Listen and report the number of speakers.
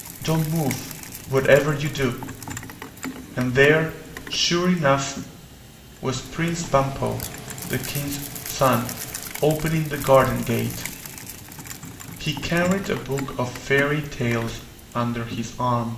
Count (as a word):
one